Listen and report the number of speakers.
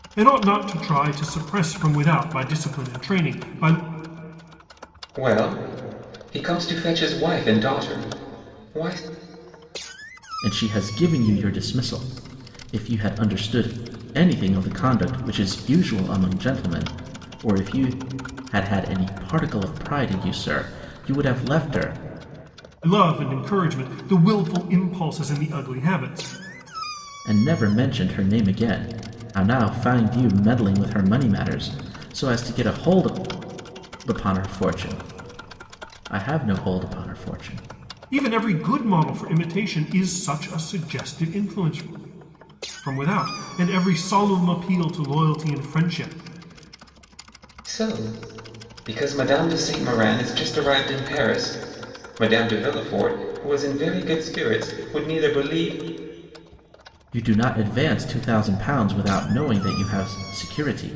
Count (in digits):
3